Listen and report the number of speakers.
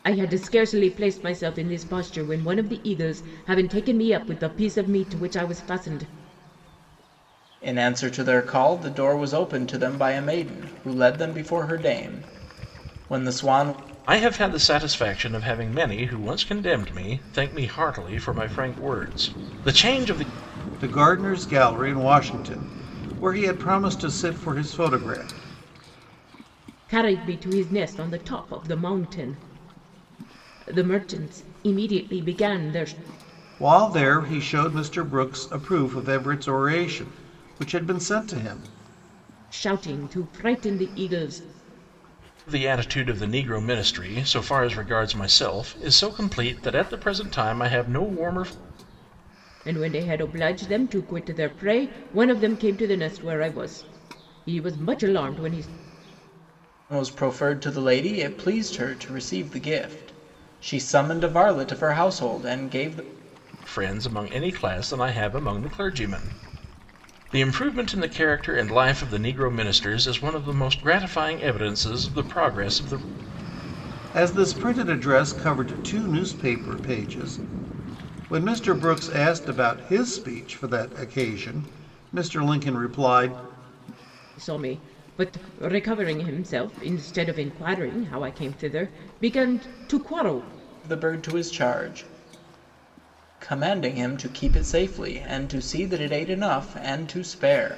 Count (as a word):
four